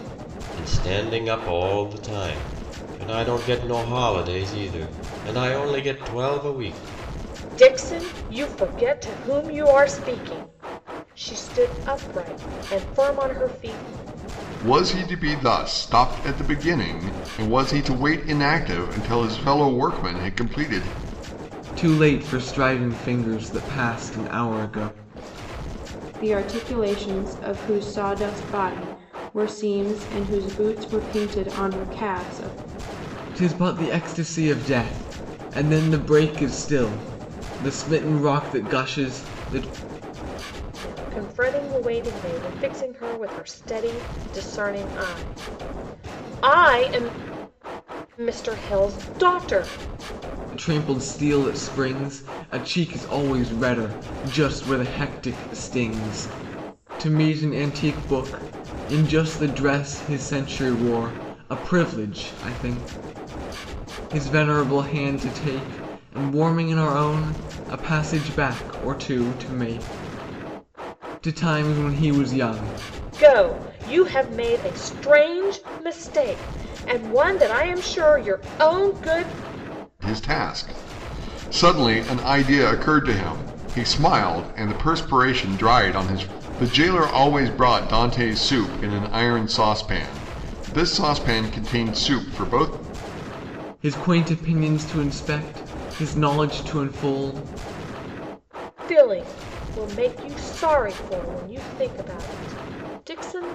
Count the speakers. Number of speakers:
5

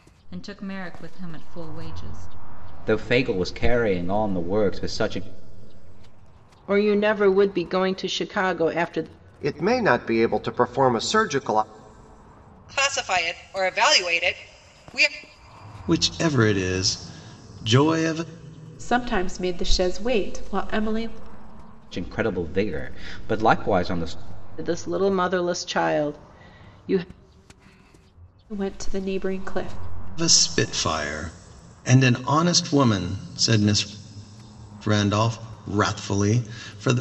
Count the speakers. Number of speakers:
7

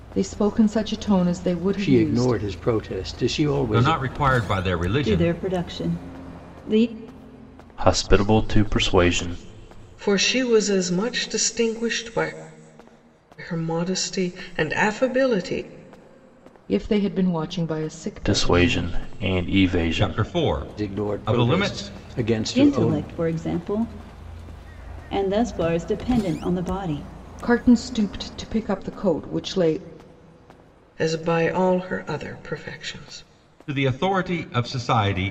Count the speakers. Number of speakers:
6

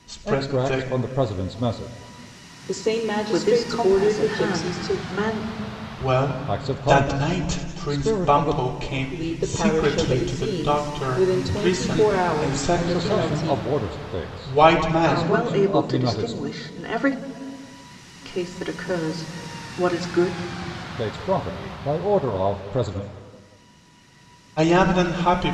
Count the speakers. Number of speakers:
4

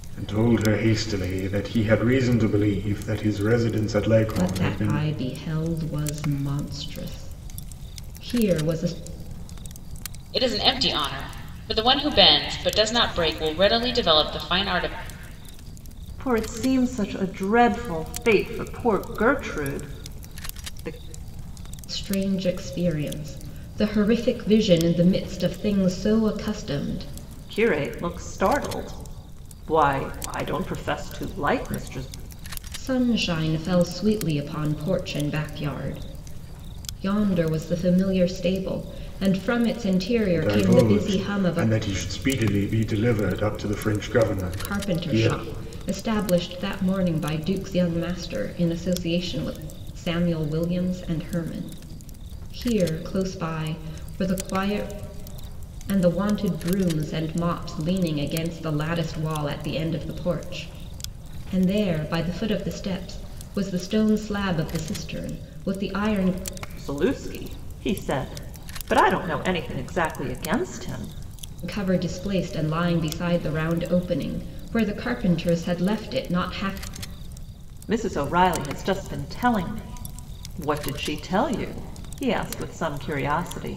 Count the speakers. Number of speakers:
4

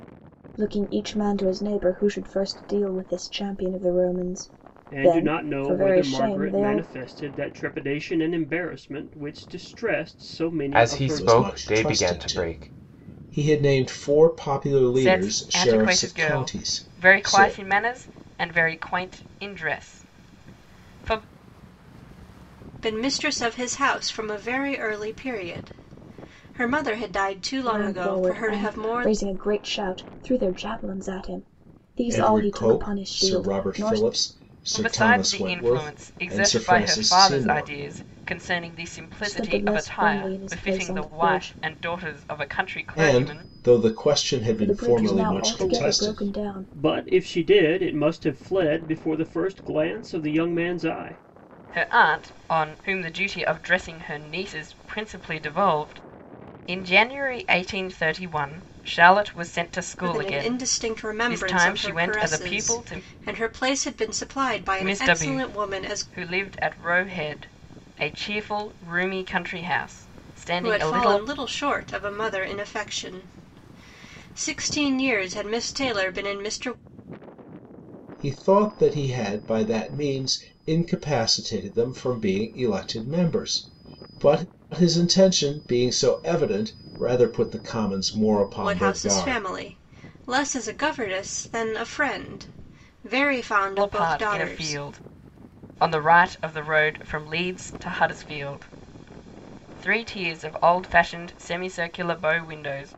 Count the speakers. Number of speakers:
6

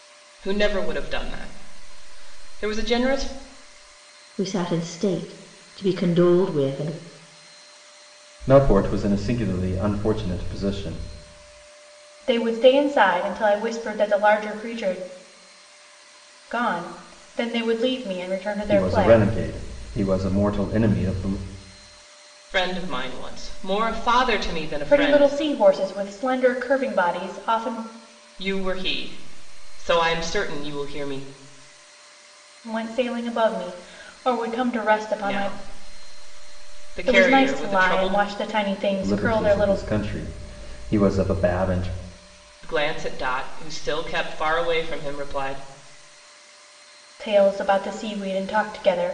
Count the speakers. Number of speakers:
4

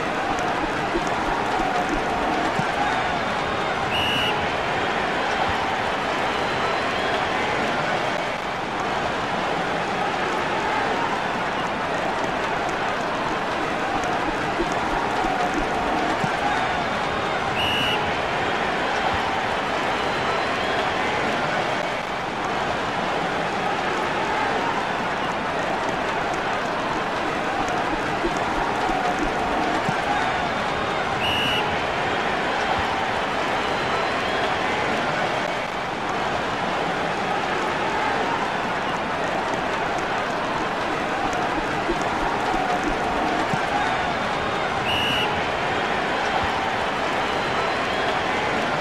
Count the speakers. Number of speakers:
0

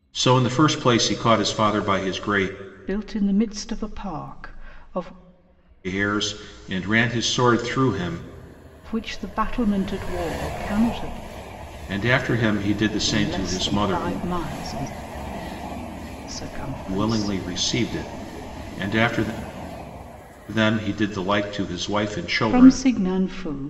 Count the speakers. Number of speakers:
2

